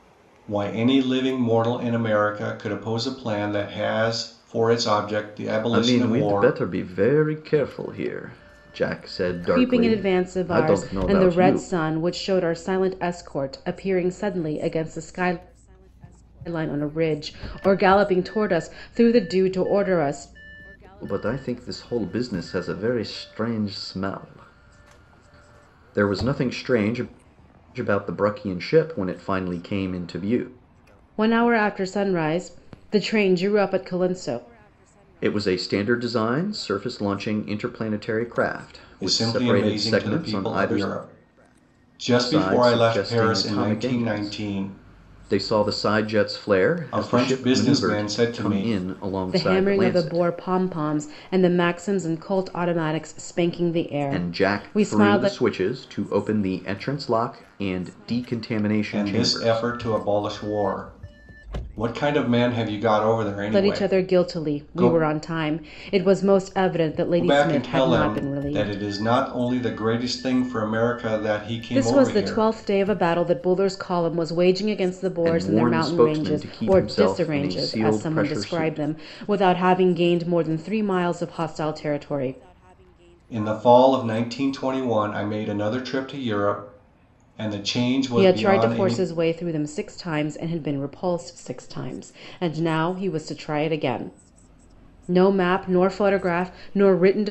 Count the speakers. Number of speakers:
3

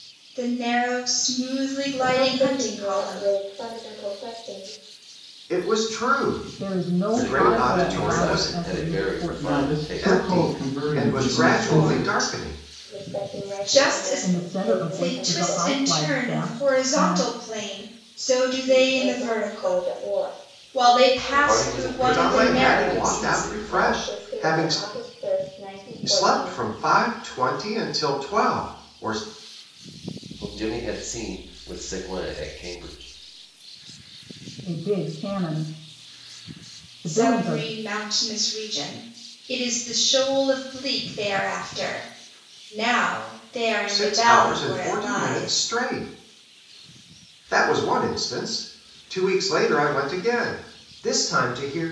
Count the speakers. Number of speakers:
6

